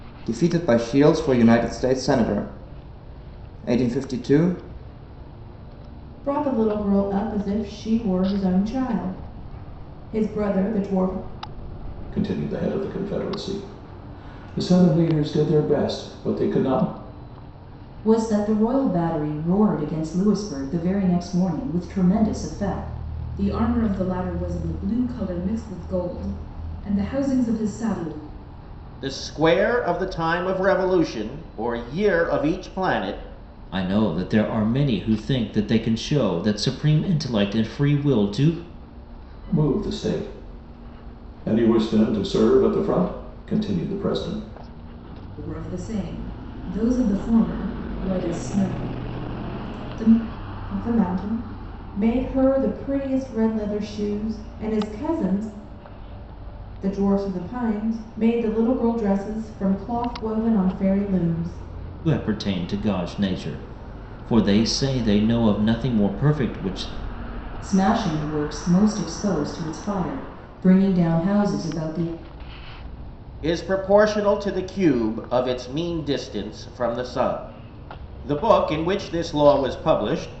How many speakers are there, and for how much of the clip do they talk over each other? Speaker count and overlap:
7, no overlap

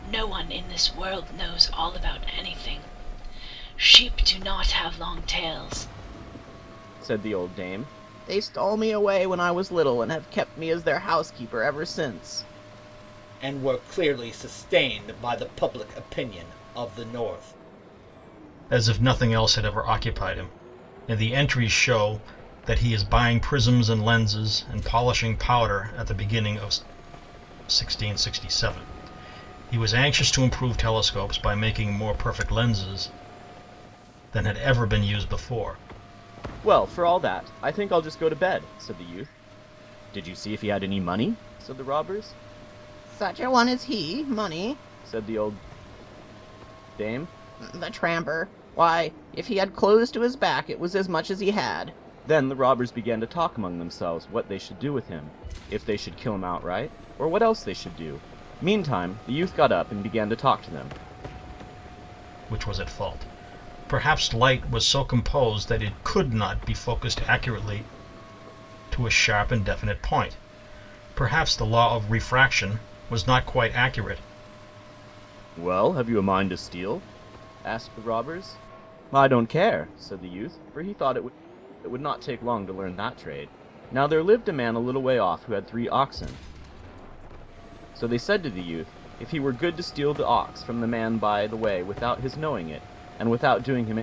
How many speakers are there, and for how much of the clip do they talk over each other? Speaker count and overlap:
4, no overlap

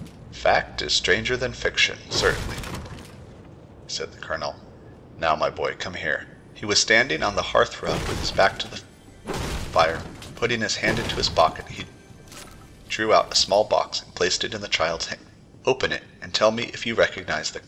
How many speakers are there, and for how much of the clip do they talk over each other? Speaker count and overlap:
1, no overlap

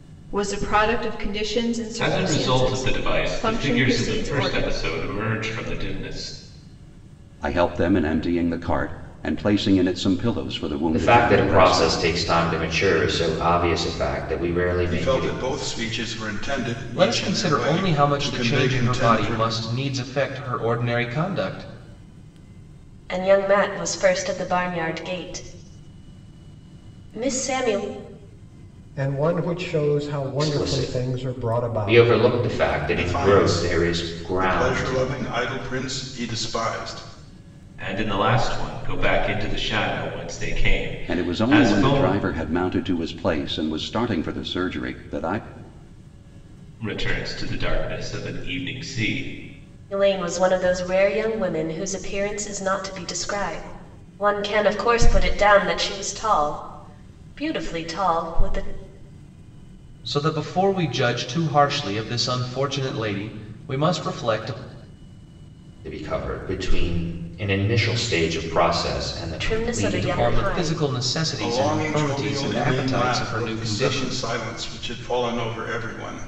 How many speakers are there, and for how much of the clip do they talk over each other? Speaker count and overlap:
8, about 22%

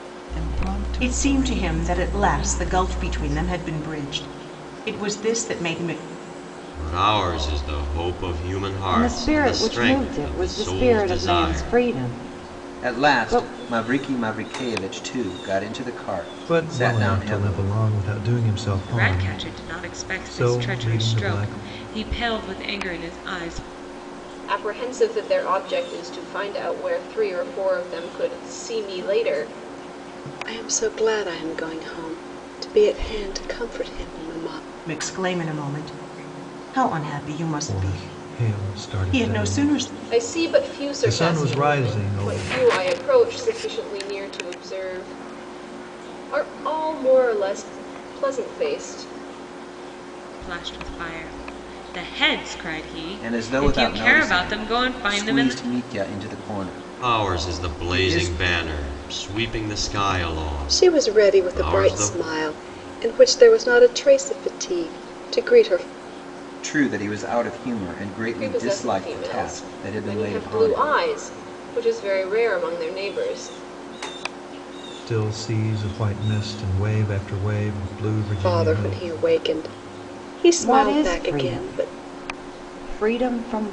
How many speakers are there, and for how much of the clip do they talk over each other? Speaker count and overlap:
9, about 30%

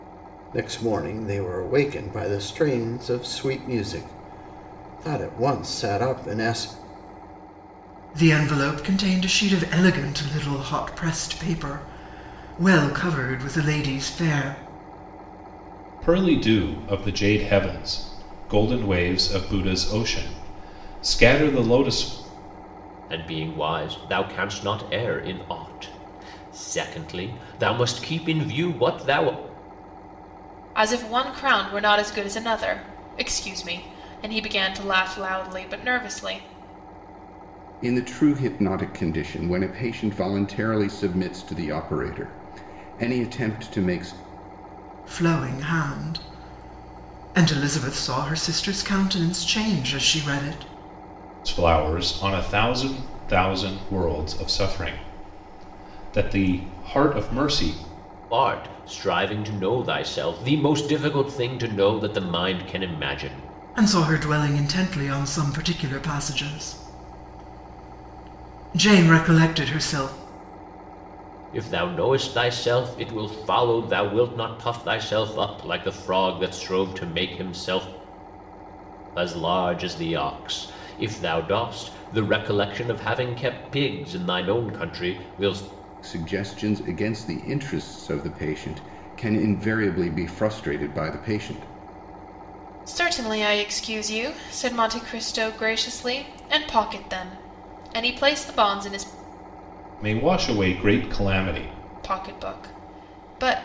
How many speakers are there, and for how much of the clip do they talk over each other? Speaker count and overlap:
6, no overlap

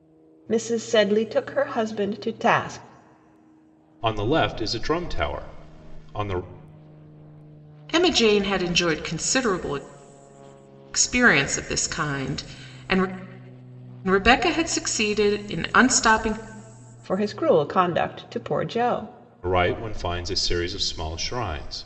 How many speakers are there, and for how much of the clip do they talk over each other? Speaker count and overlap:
3, no overlap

